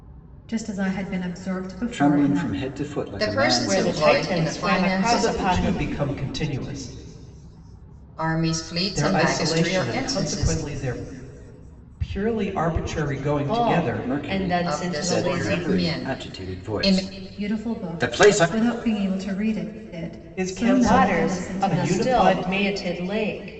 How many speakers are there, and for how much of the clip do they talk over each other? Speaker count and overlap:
5, about 51%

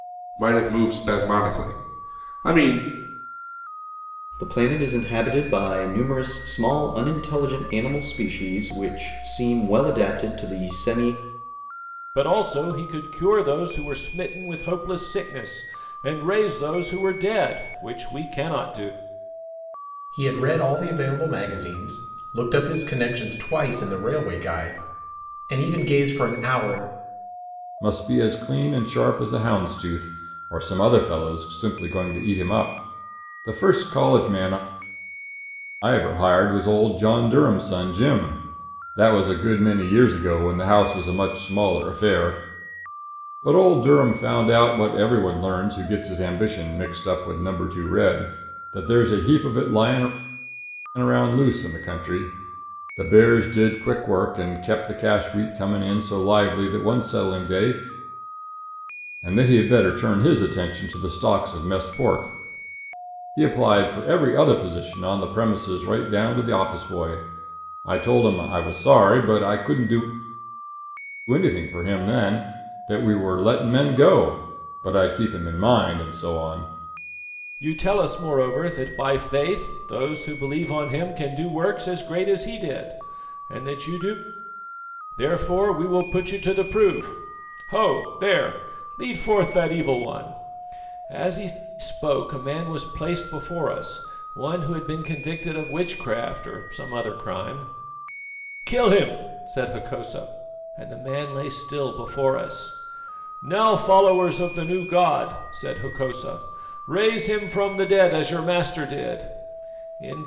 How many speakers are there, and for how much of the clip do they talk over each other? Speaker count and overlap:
5, no overlap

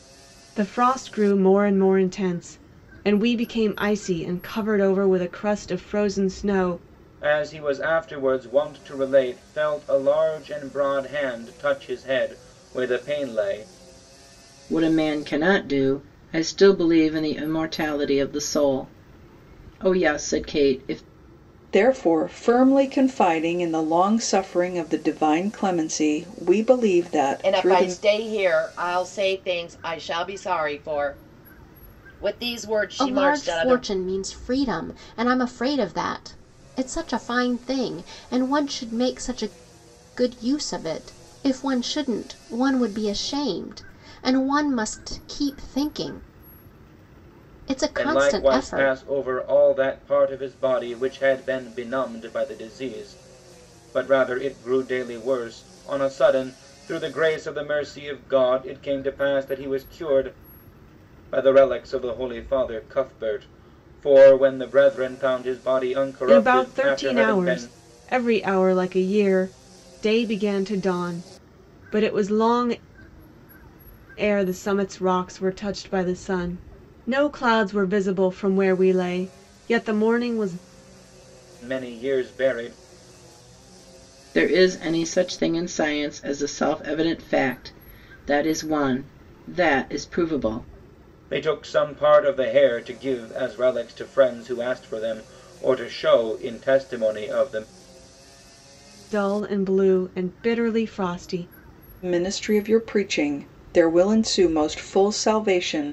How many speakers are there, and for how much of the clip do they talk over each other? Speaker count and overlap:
6, about 4%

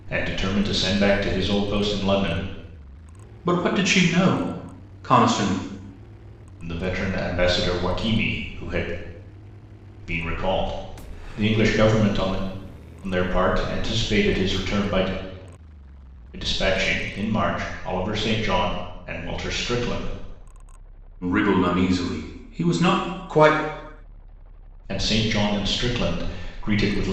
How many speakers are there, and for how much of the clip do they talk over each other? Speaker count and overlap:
2, no overlap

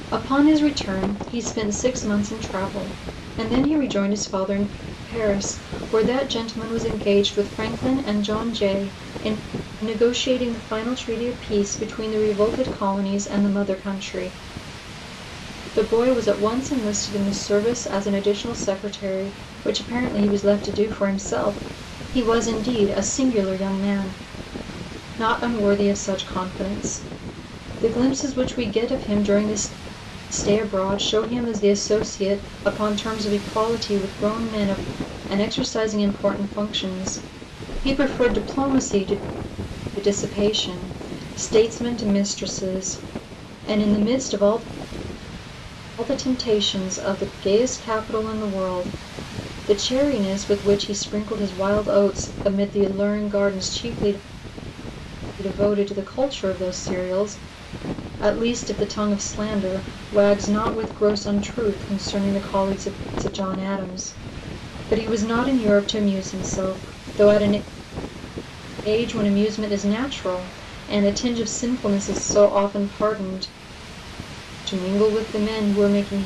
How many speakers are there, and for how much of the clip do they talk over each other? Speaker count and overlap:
1, no overlap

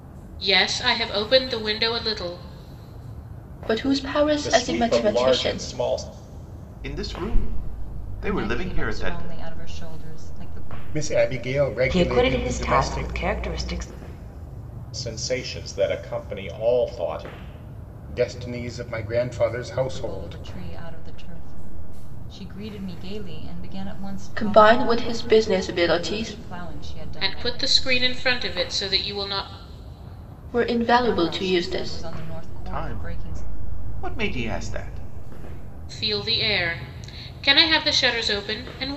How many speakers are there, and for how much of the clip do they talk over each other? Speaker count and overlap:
7, about 20%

